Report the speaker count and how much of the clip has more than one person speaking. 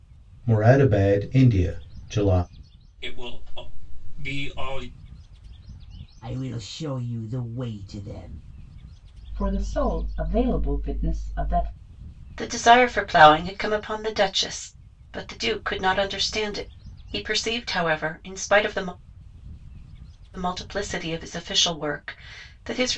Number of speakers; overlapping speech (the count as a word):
five, no overlap